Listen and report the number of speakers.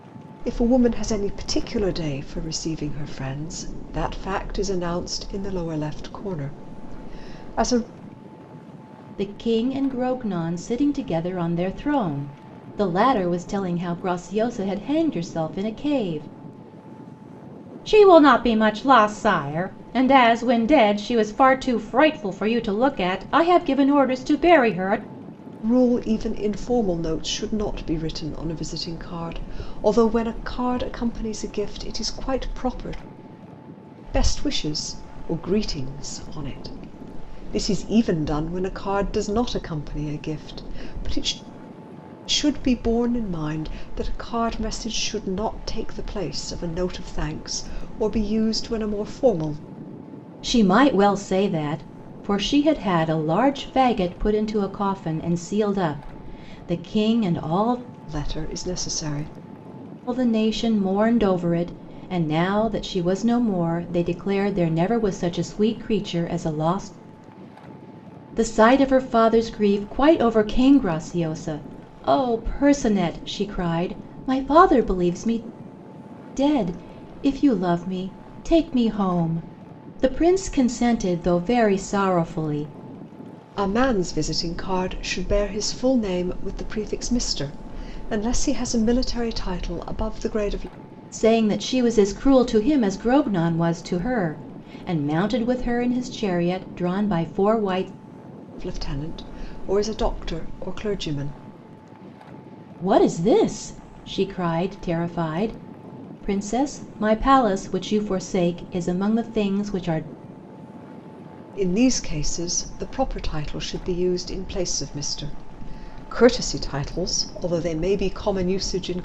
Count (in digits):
2